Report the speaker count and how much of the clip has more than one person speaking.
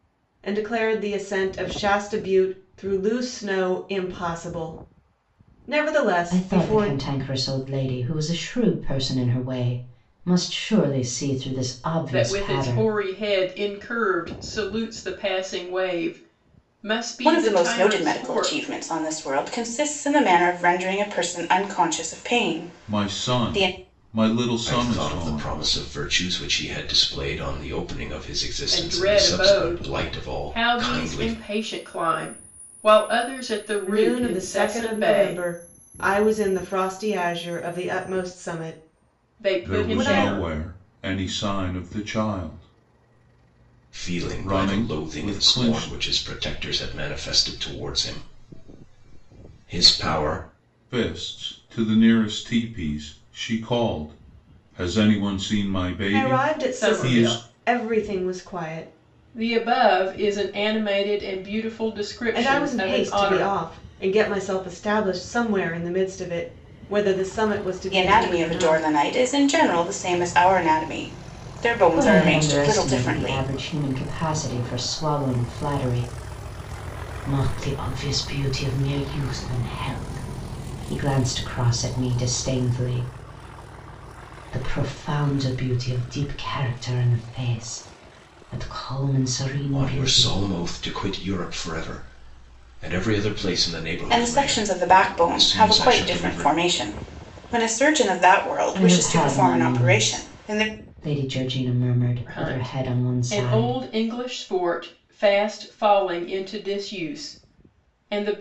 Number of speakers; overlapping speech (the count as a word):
six, about 23%